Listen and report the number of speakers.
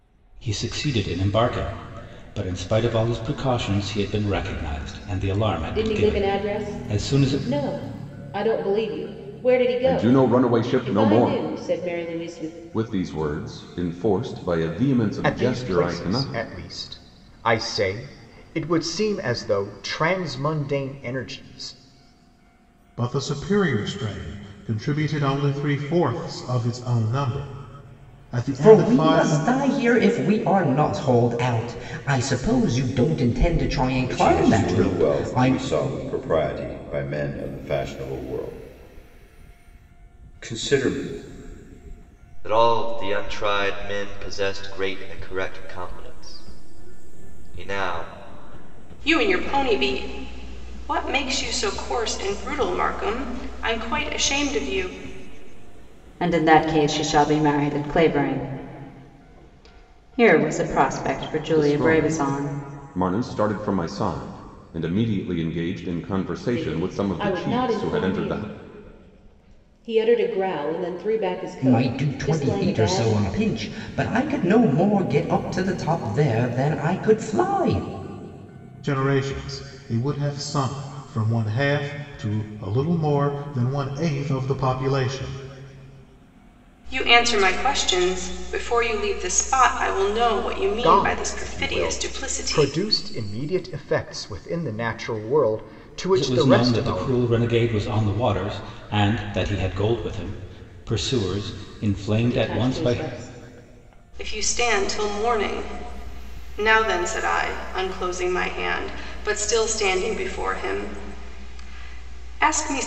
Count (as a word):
ten